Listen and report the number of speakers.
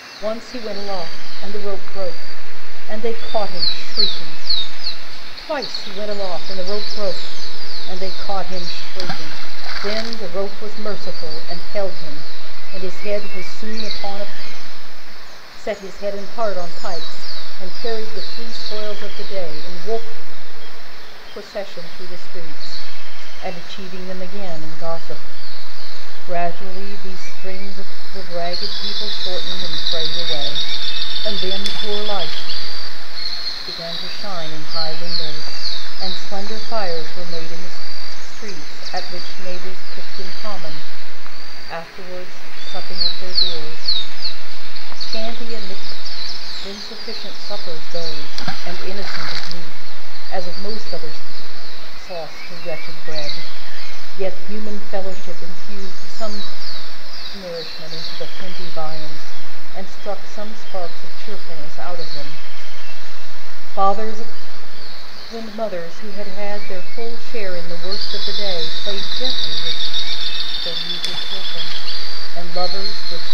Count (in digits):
1